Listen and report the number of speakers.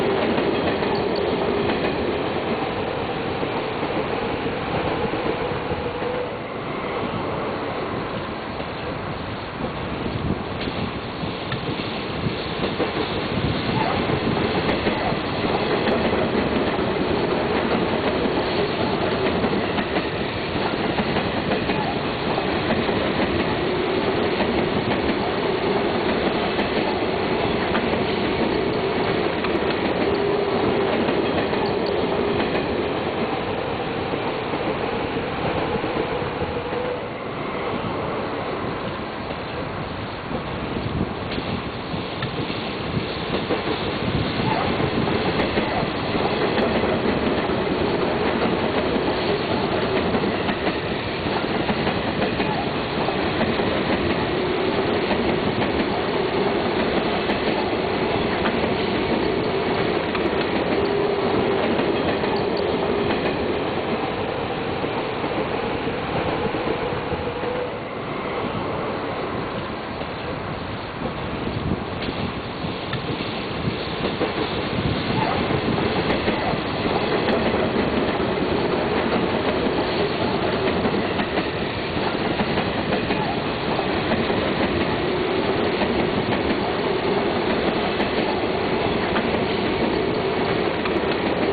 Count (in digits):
0